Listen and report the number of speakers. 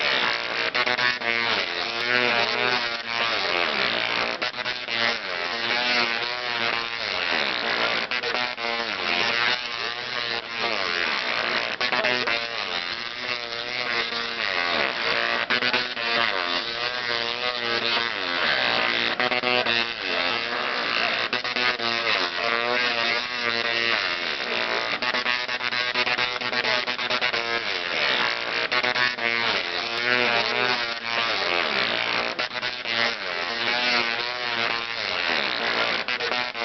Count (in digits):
0